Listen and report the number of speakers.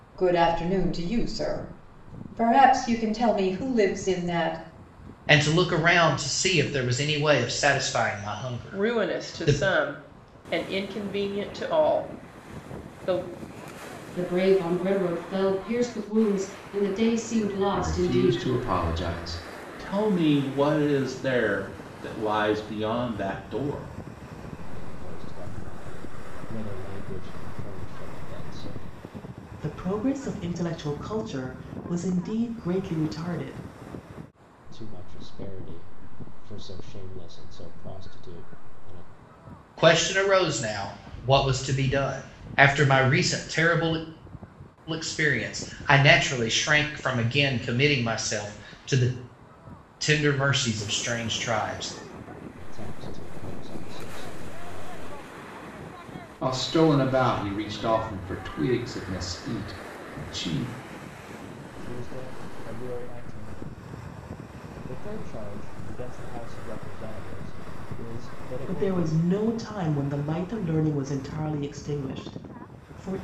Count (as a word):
eight